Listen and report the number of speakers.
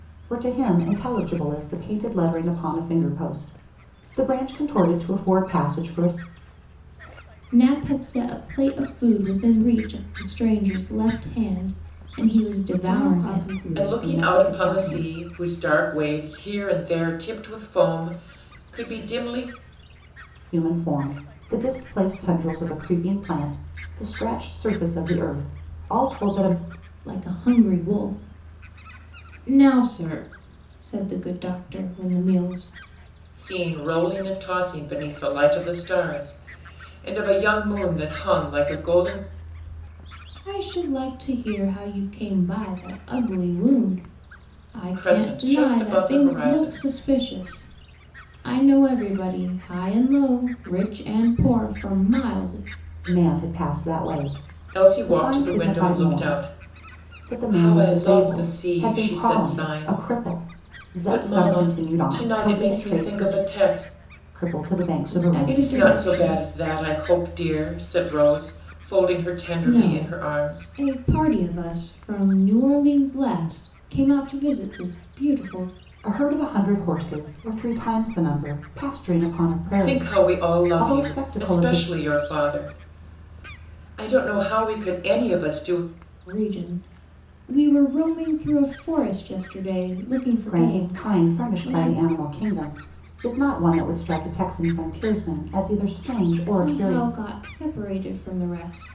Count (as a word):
four